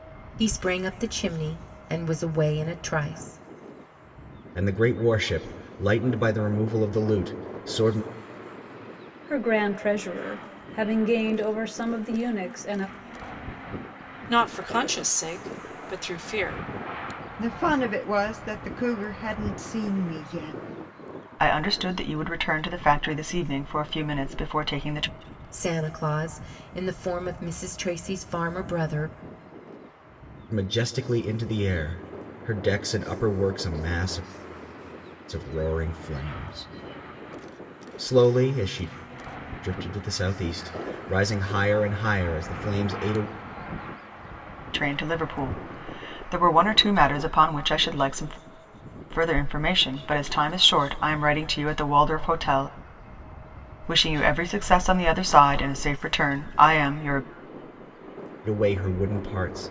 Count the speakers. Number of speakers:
6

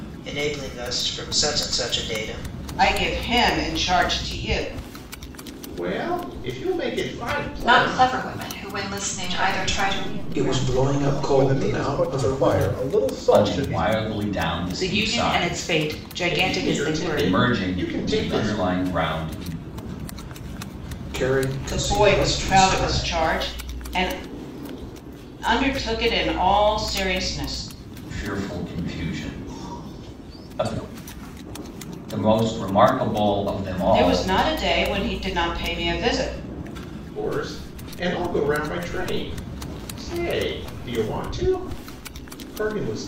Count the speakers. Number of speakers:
9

